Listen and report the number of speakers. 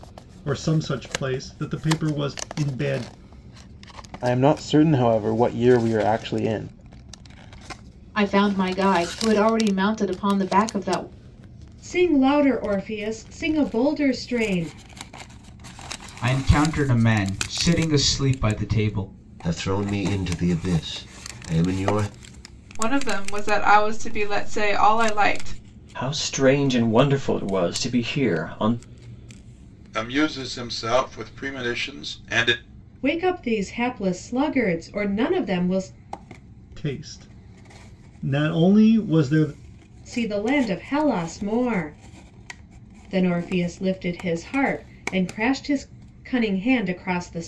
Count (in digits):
9